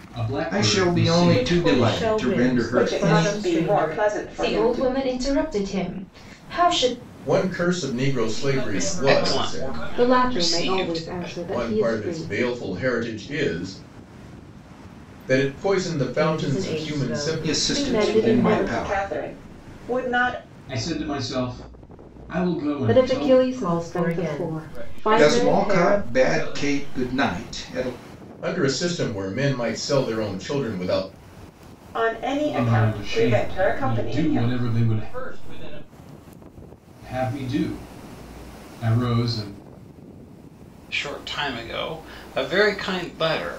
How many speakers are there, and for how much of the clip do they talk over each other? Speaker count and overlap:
9, about 41%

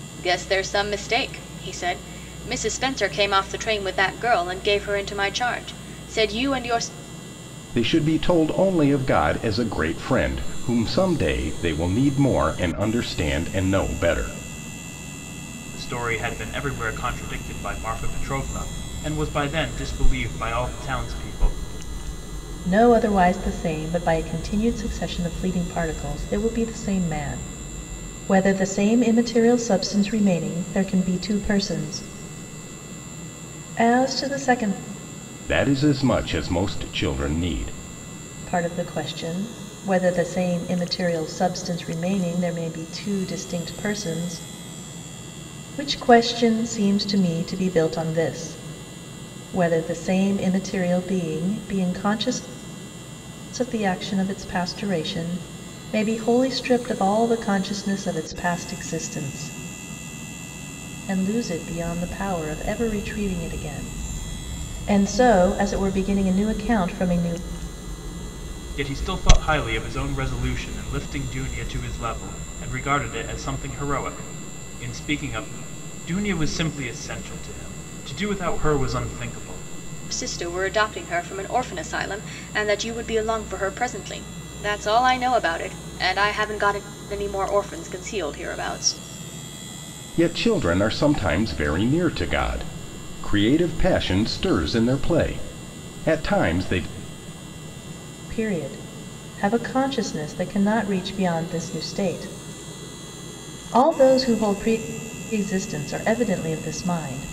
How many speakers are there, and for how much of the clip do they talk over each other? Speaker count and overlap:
4, no overlap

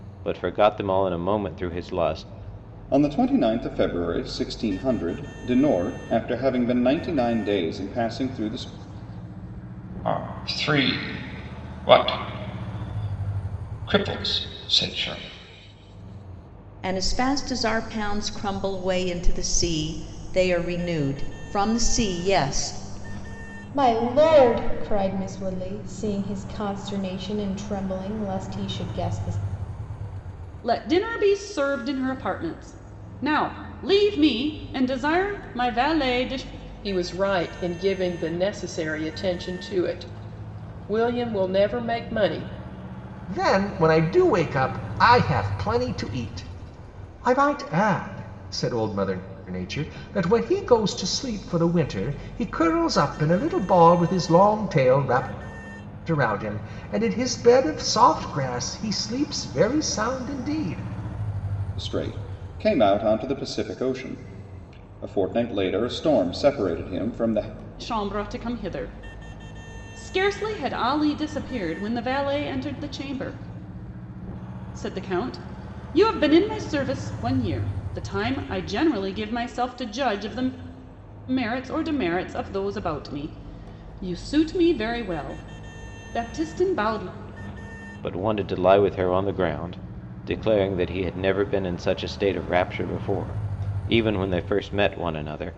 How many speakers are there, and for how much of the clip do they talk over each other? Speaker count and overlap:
8, no overlap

